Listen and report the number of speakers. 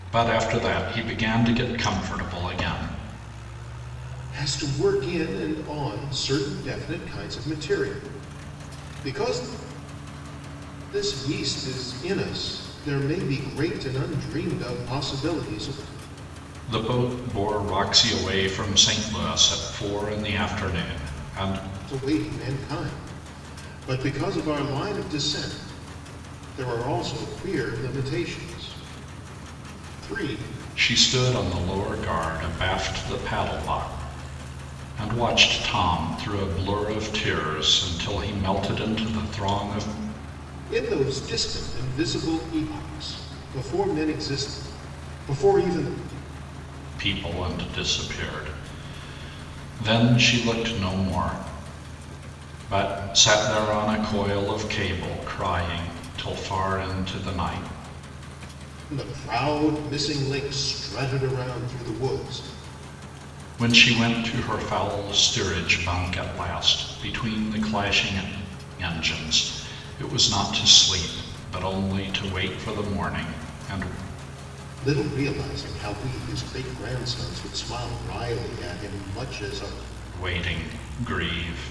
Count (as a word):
two